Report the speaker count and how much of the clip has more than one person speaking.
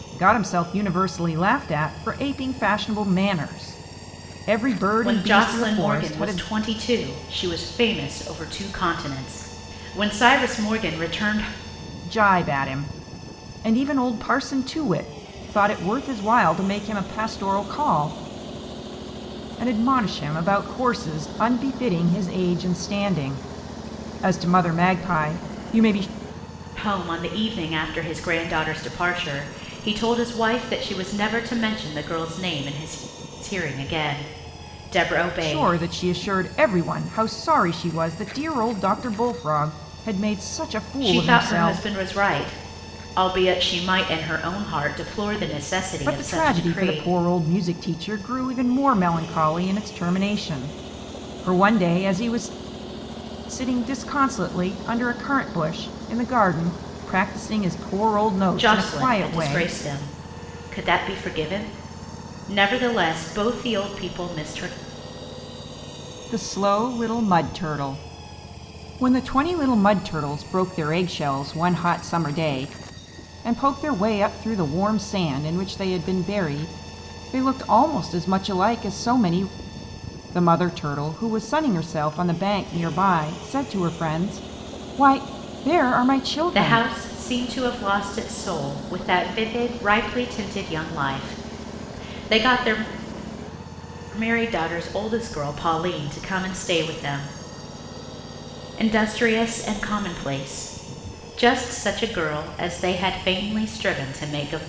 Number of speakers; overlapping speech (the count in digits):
2, about 5%